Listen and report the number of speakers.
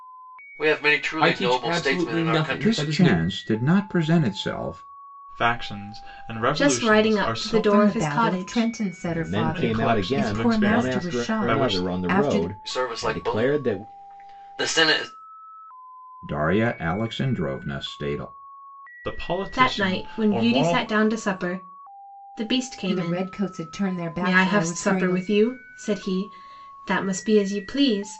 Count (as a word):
seven